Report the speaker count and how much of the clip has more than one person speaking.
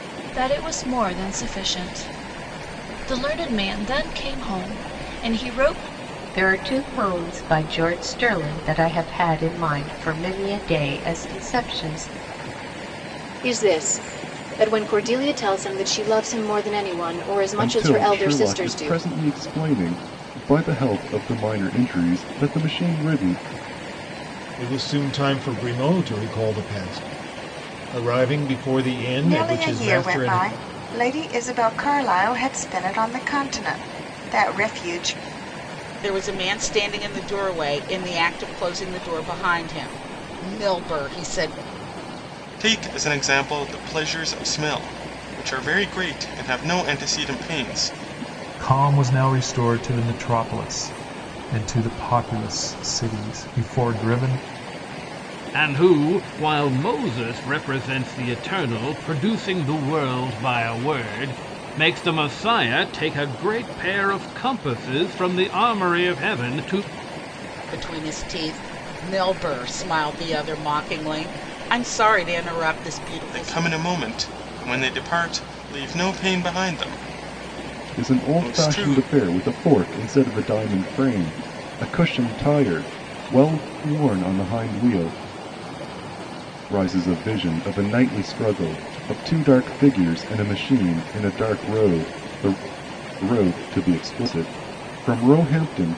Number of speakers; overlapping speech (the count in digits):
10, about 4%